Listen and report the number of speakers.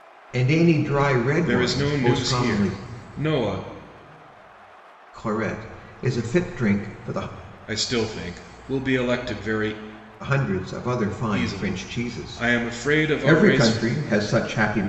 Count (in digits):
2